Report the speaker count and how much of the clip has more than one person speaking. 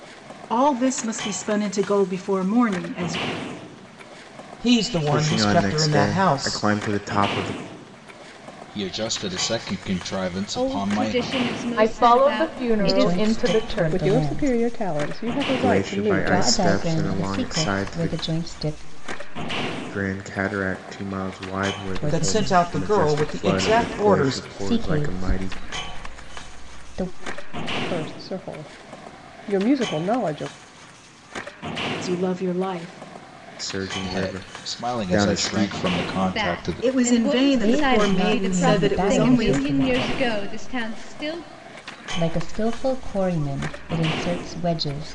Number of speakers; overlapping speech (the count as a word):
eight, about 38%